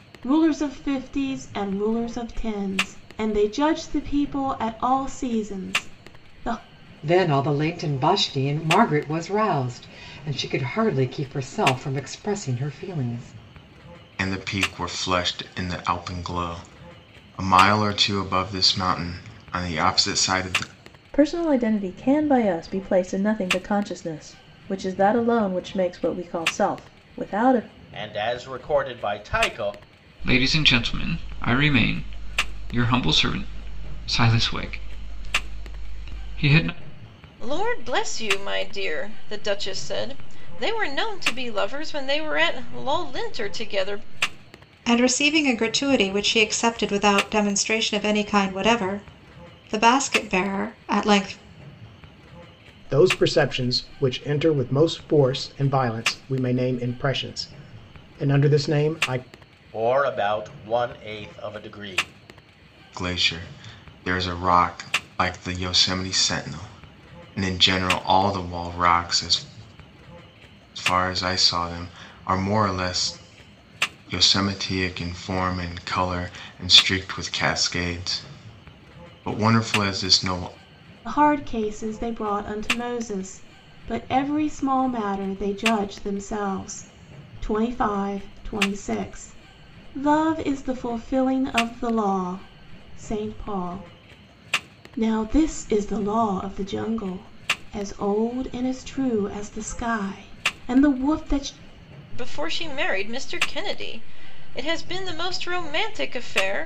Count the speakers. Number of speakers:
9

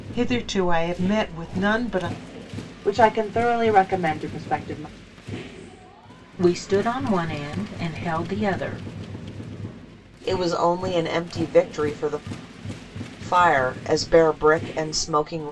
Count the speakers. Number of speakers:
4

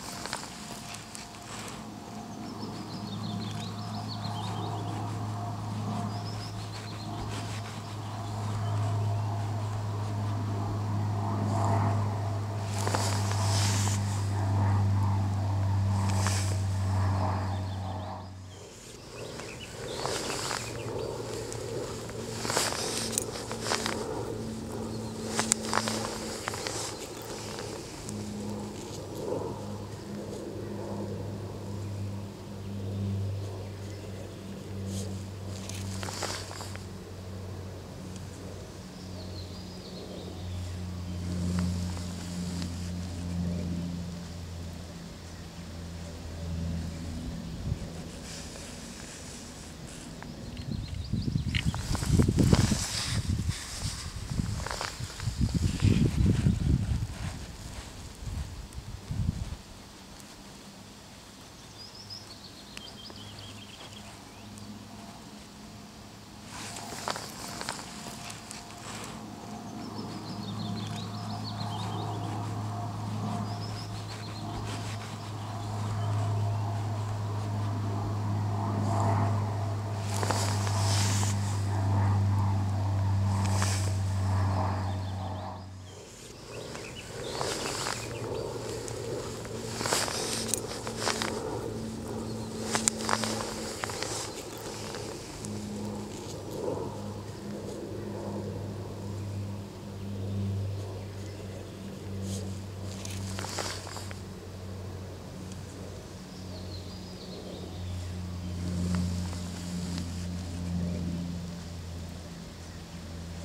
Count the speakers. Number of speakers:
0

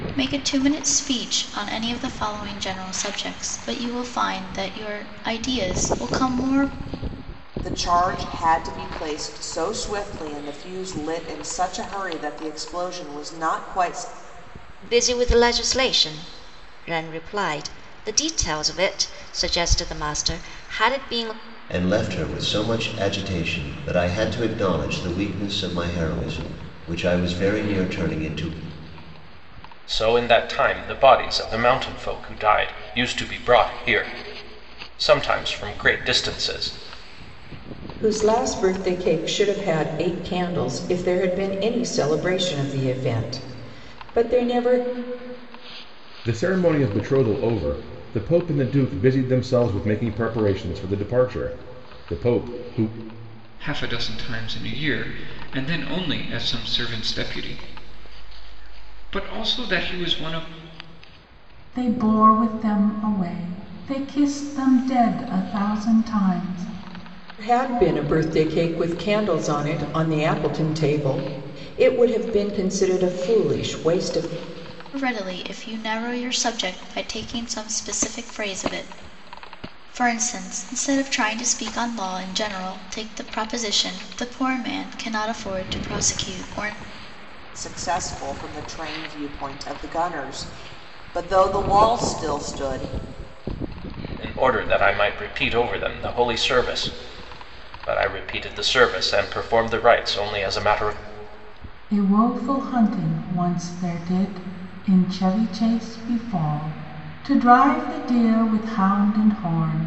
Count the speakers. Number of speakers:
9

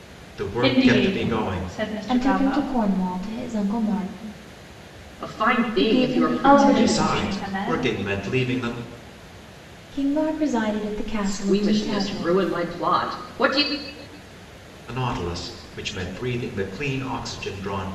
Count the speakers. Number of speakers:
4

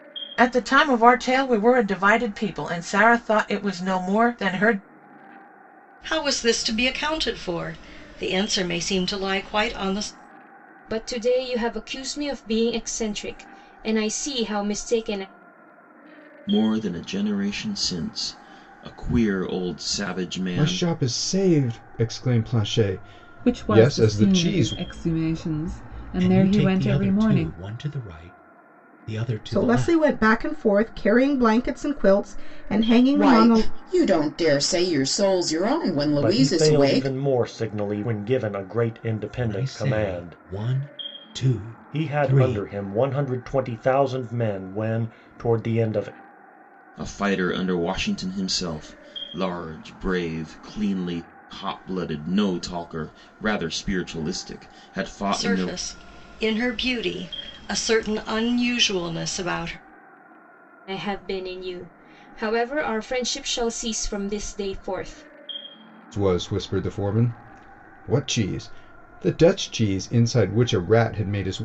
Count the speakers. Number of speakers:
10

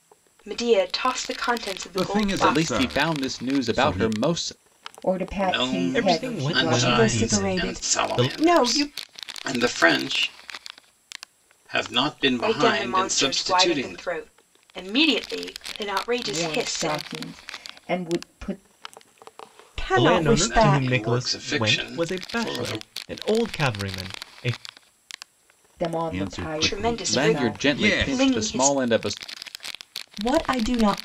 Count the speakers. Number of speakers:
7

